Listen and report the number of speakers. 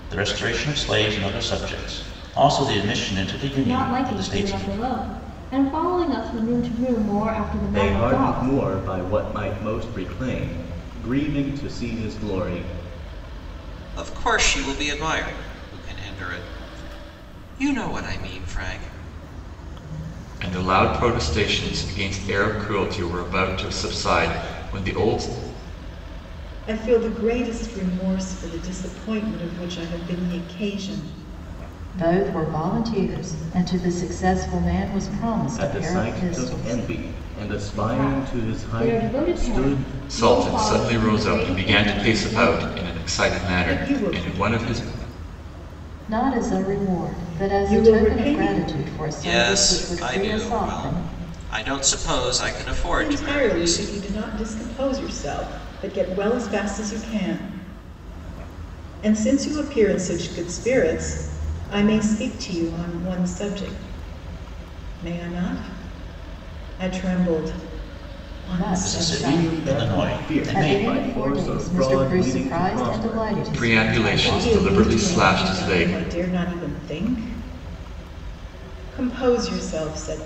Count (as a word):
seven